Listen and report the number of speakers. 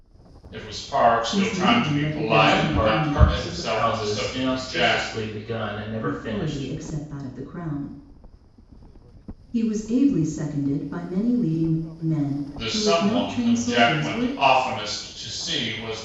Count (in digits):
3